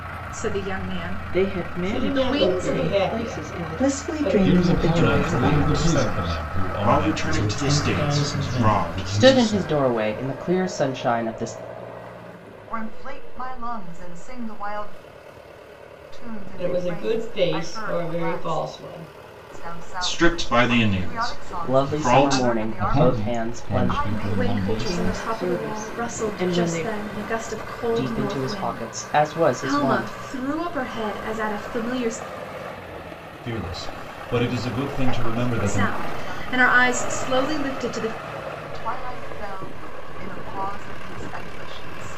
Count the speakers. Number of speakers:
10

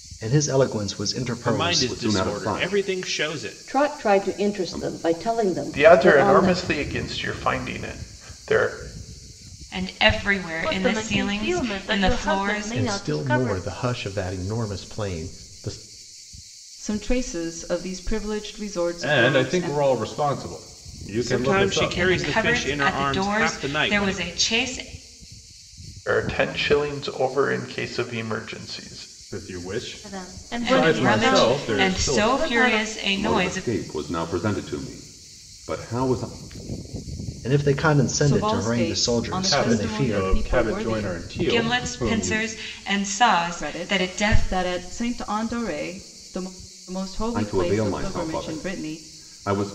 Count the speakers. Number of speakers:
10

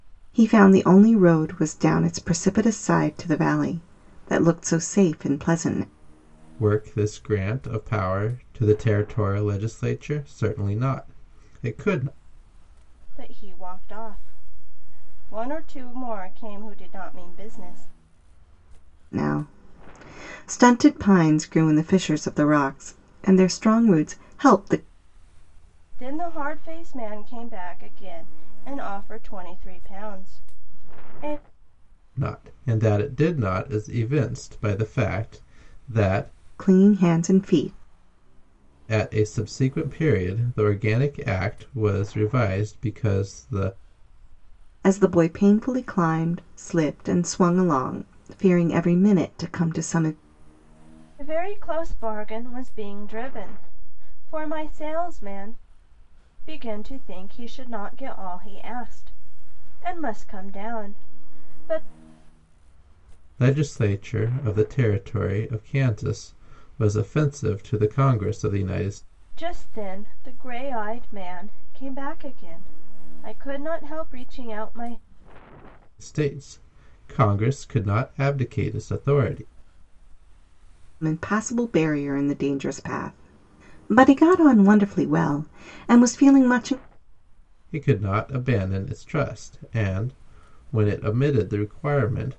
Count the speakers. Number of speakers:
3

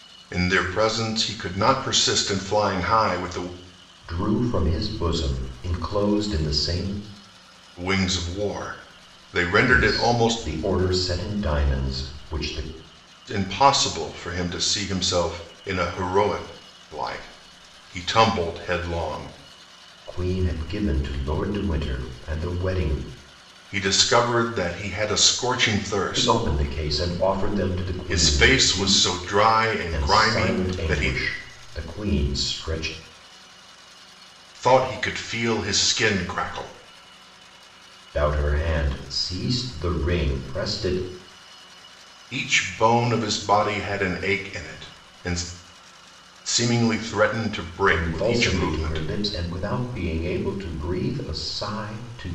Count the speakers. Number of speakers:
2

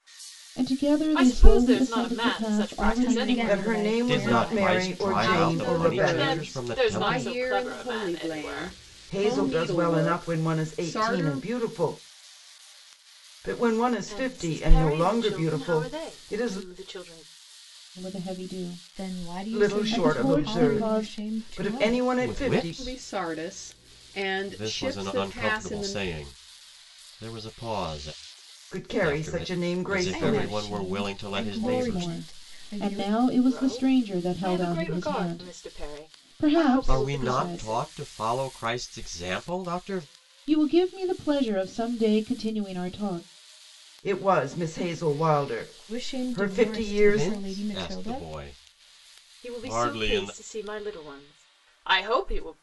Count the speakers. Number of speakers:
6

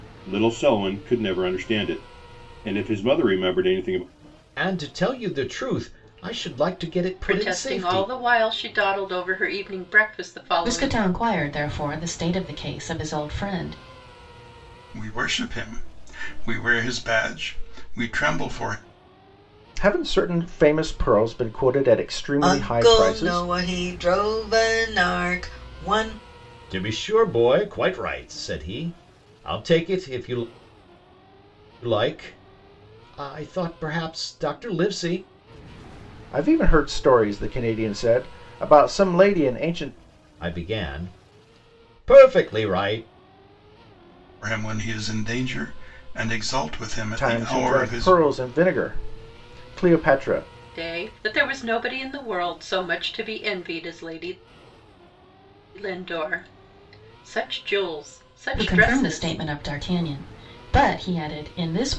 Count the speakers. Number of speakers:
7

